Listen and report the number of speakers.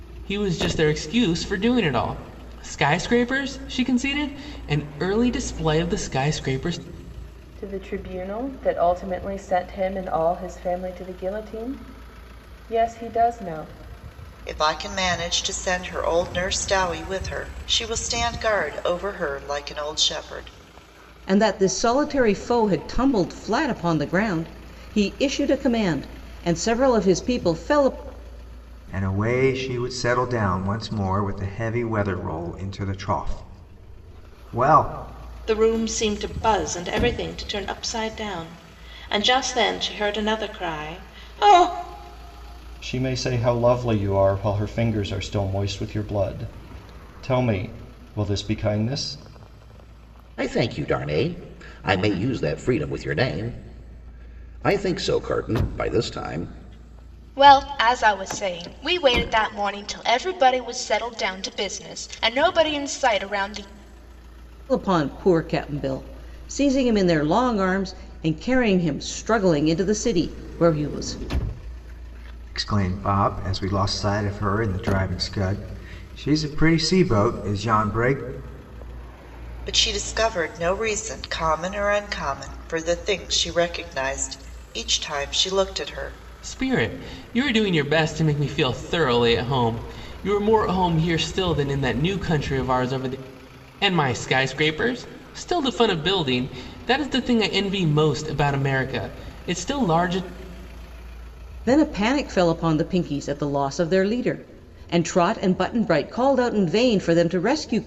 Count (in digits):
9